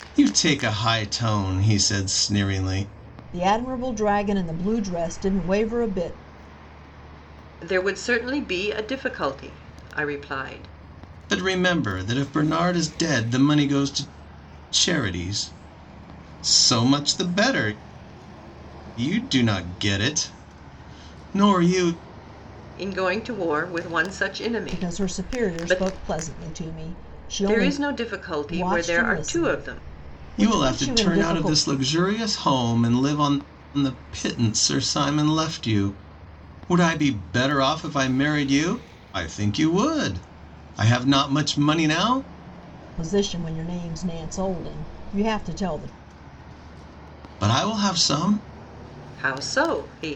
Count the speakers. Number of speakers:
3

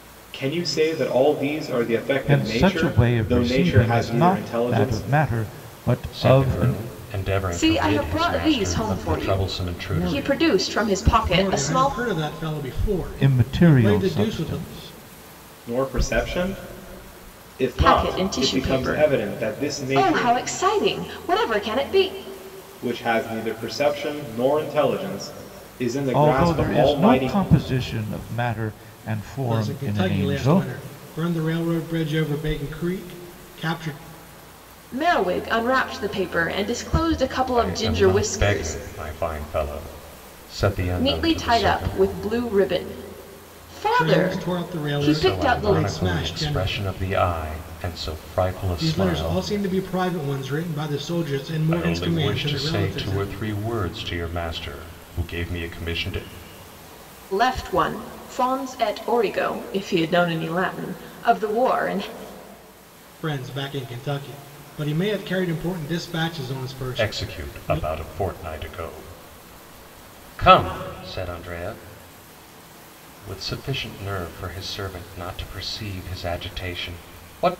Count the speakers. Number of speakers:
5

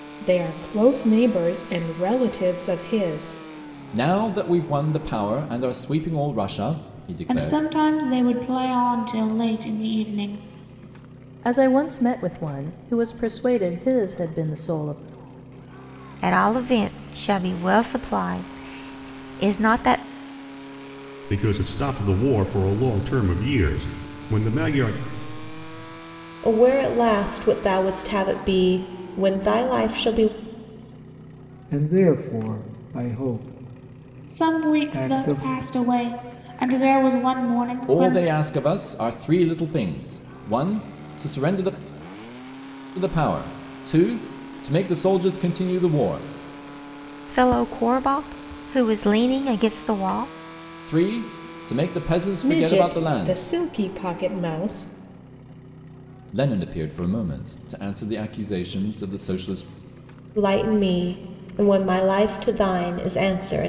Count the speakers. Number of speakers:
8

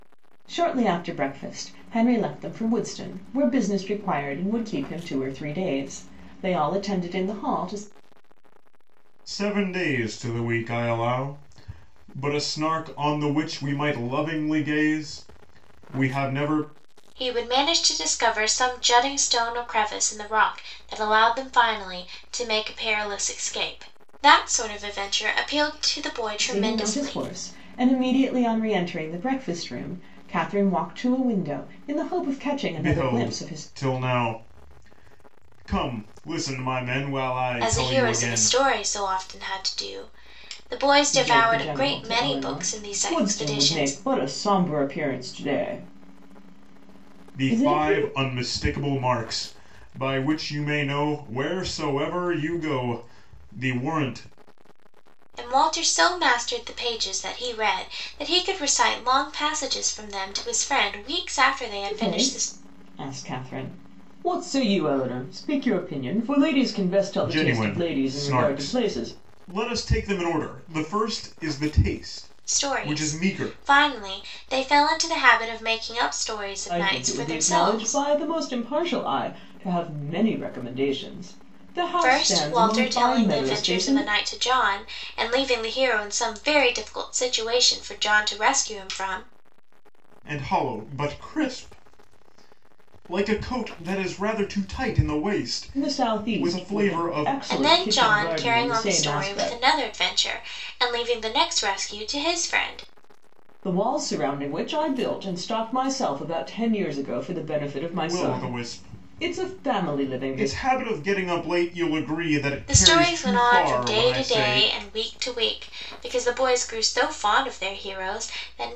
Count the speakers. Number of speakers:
3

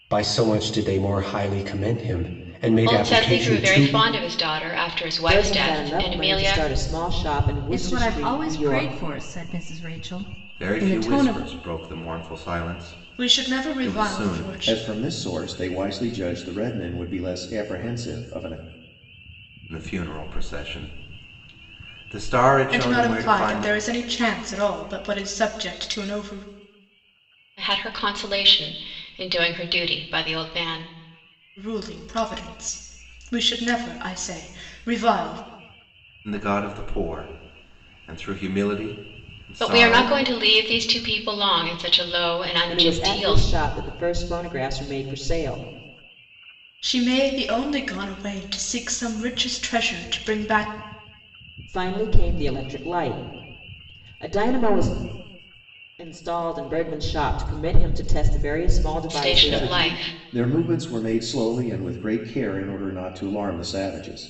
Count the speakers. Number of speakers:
7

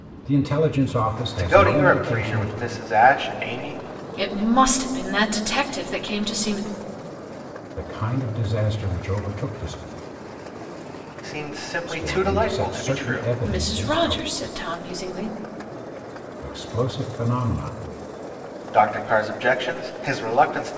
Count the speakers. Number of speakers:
3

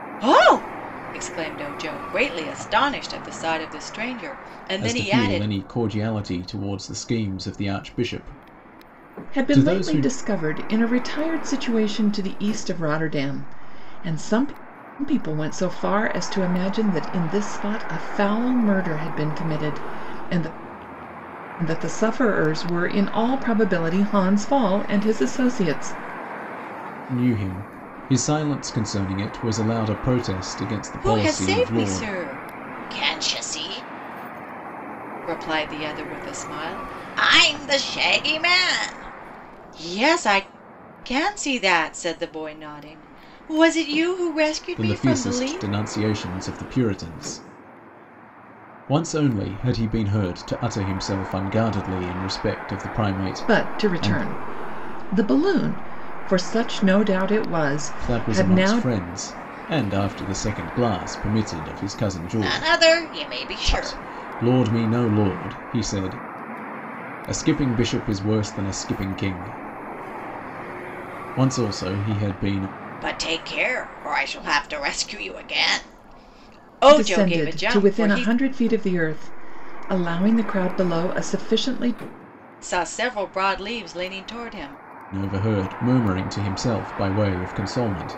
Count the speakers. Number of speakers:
3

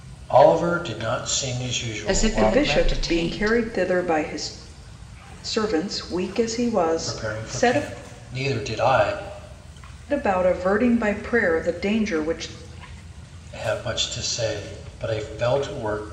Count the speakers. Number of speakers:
3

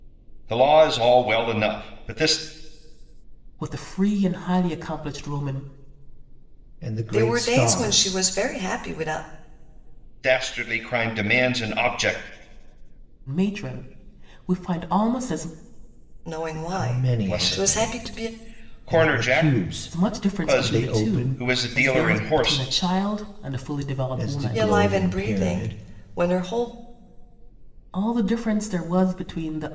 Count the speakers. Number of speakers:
4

